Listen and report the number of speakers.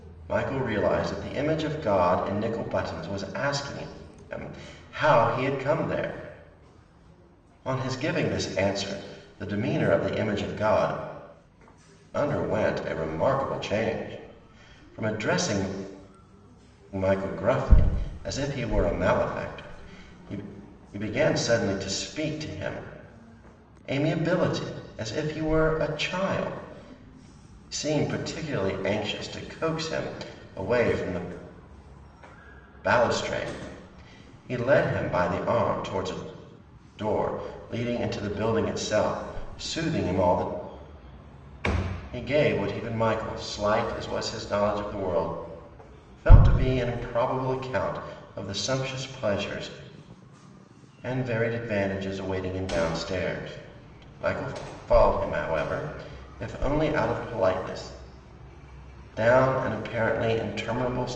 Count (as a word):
one